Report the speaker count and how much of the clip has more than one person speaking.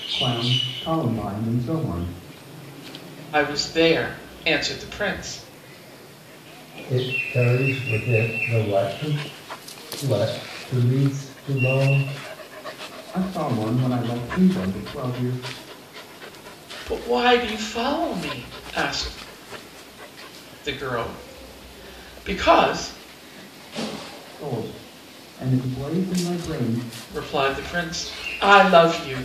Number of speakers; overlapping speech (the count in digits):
3, no overlap